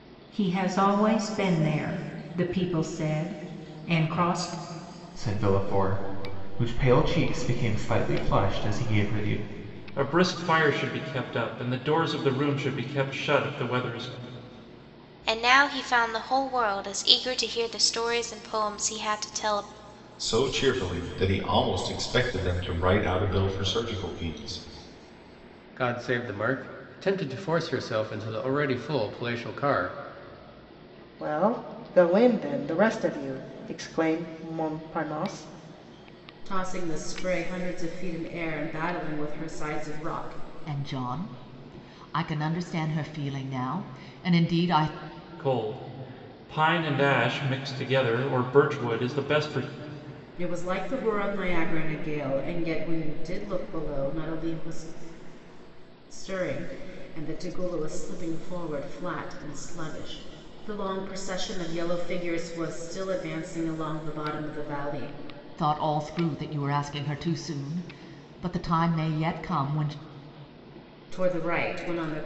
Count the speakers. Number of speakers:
nine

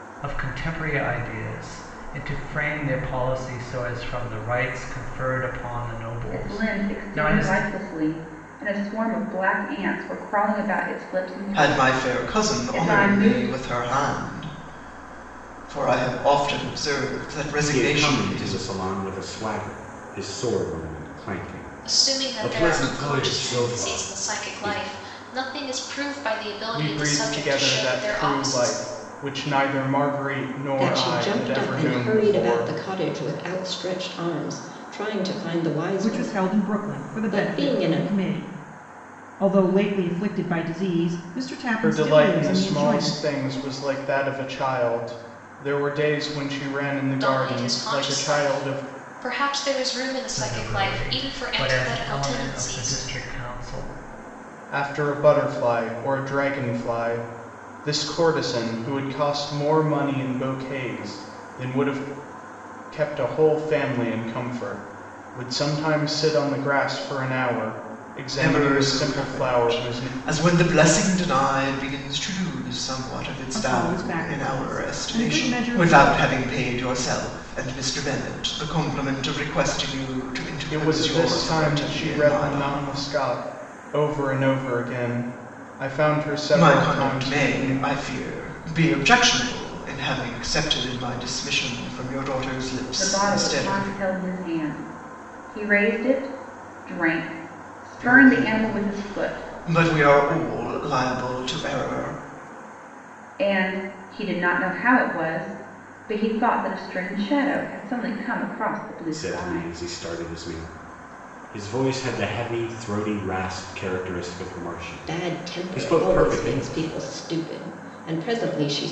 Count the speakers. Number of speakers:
eight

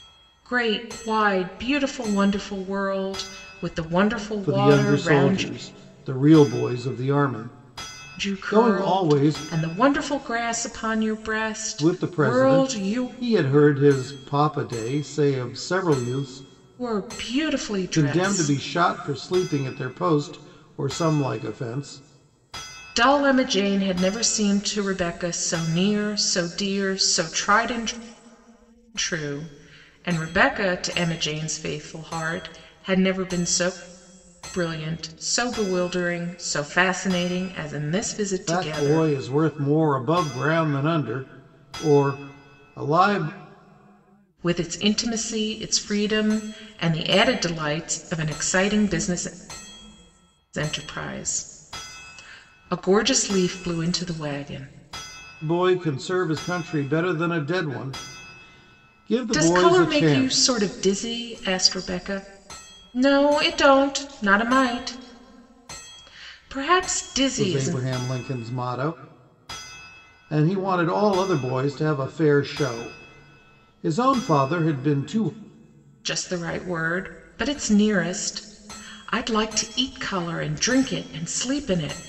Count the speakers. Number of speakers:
two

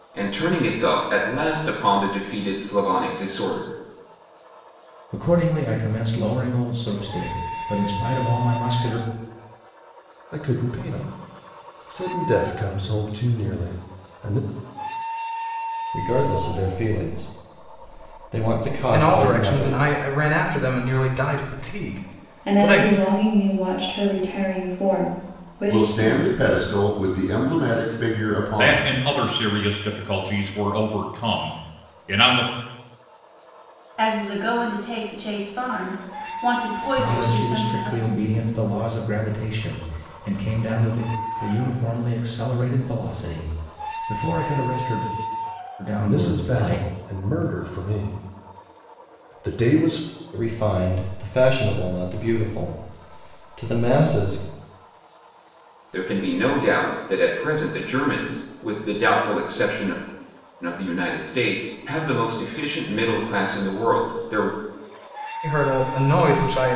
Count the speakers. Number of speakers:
nine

